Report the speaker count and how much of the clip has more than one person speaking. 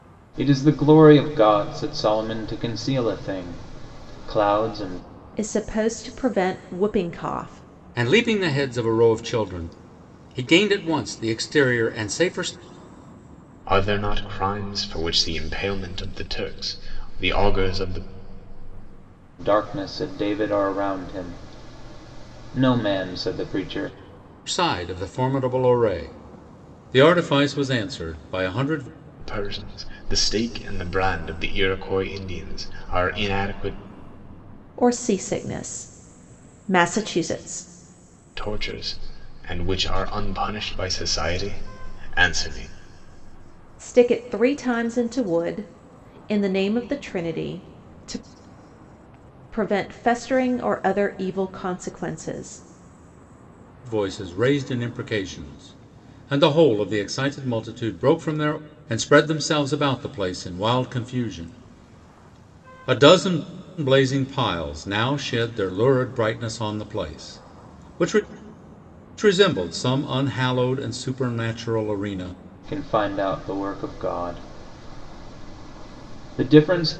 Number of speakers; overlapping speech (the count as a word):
four, no overlap